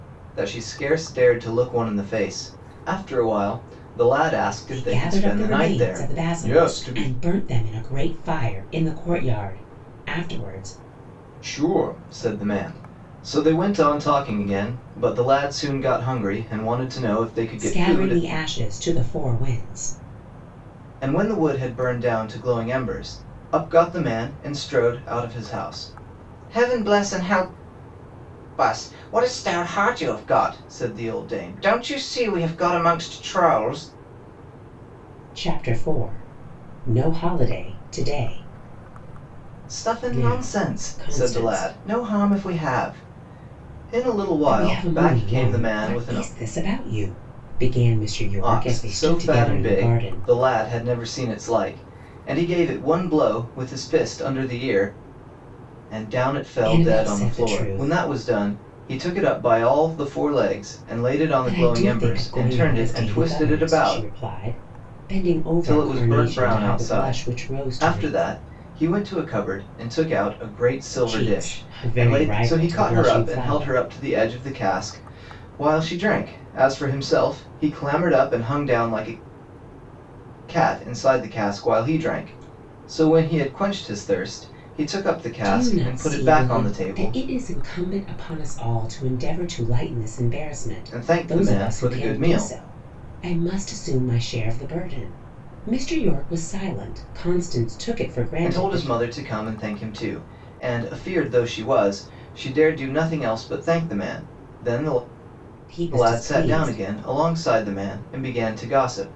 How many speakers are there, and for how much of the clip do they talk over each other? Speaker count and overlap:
2, about 21%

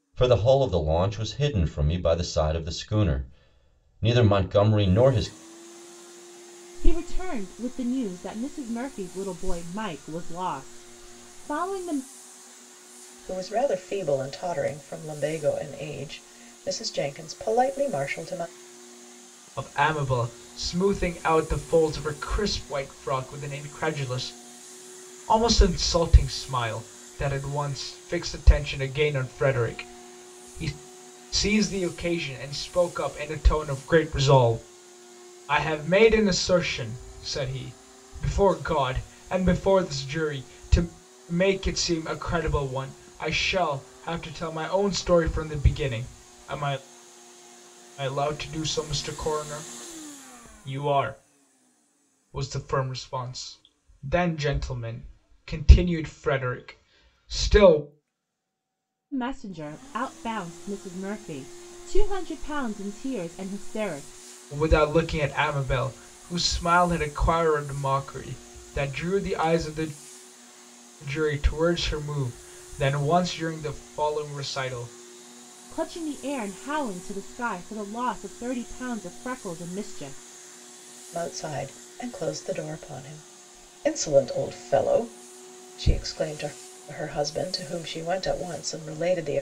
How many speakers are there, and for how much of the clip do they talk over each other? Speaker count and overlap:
4, no overlap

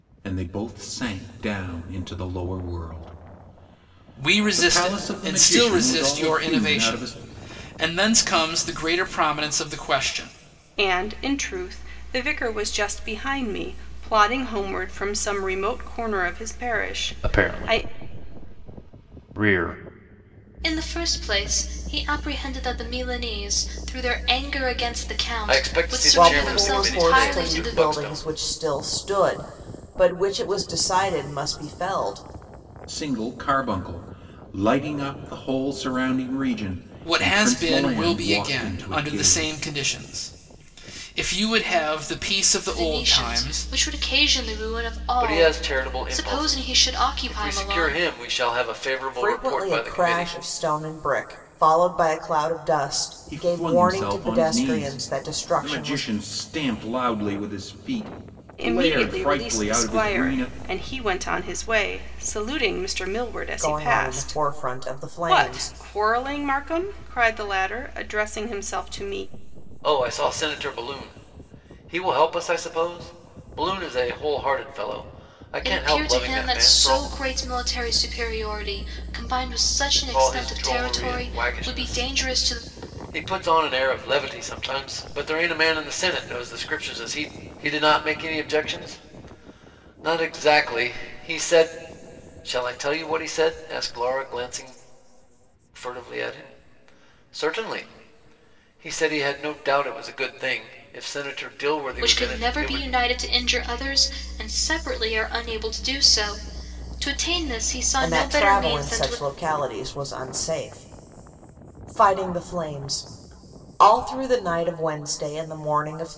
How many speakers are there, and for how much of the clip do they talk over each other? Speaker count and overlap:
7, about 23%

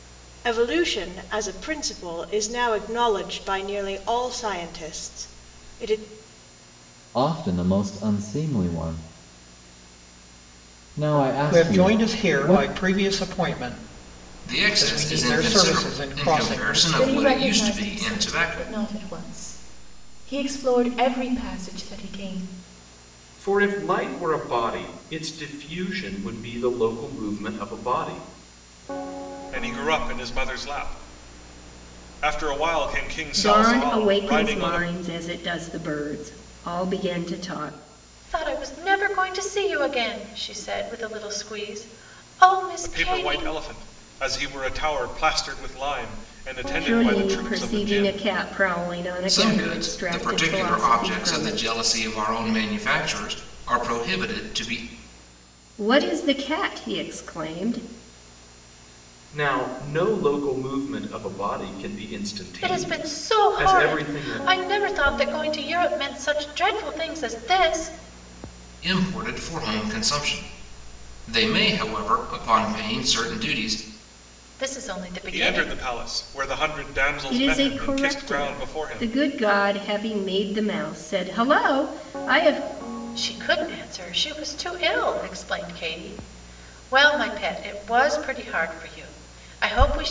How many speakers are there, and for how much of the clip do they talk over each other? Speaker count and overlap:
9, about 18%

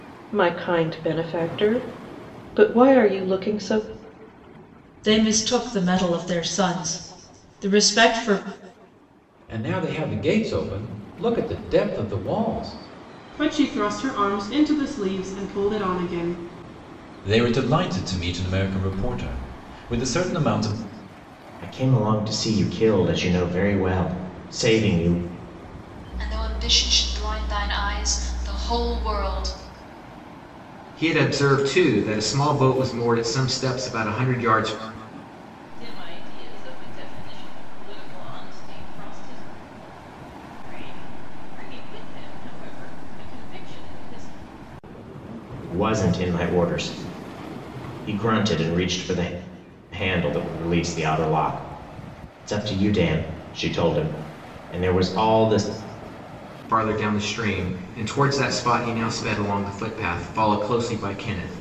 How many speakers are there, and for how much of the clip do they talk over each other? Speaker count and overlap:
9, no overlap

